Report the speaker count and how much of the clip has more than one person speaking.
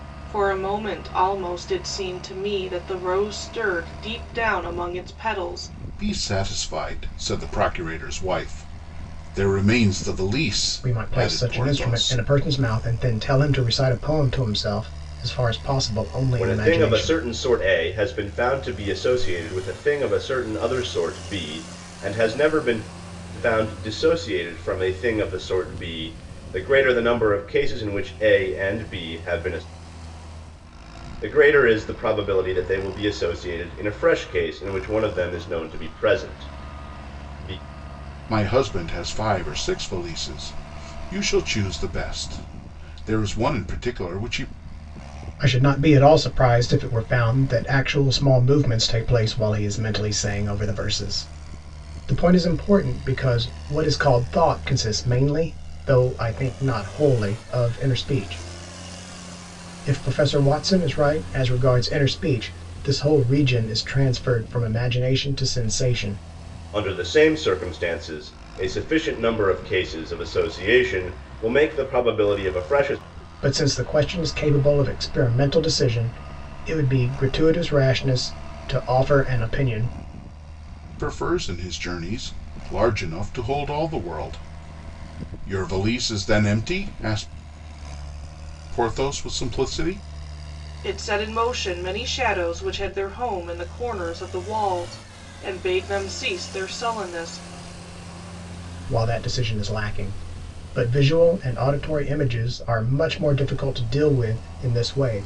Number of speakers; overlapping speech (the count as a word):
four, about 2%